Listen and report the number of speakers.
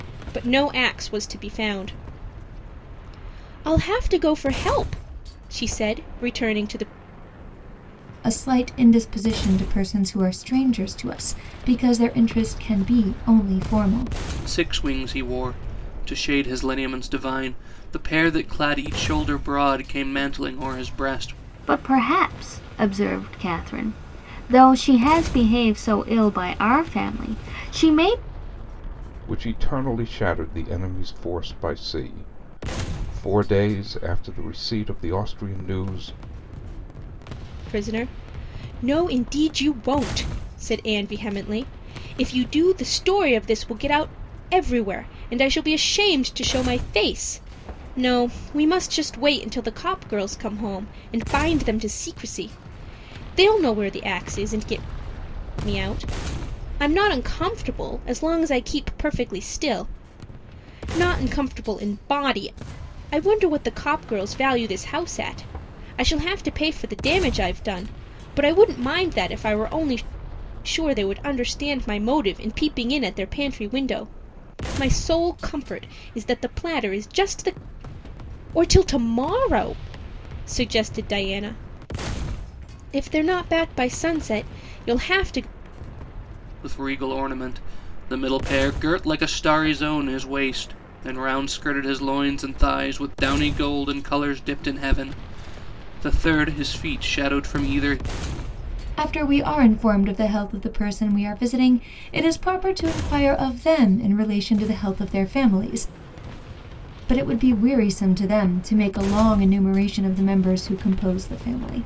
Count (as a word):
five